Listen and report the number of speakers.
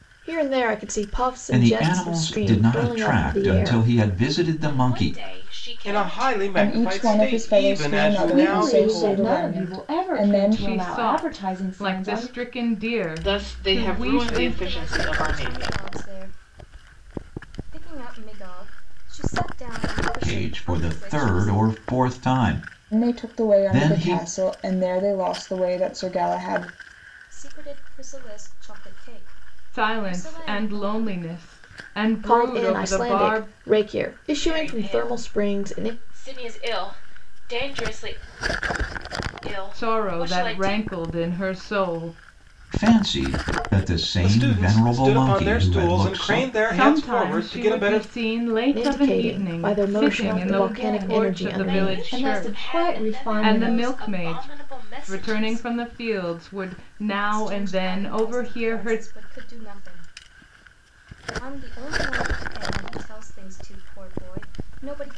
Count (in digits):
9